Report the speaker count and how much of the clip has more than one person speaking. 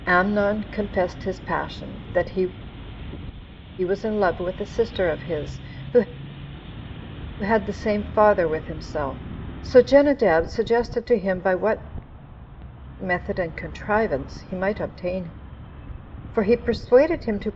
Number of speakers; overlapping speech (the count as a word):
one, no overlap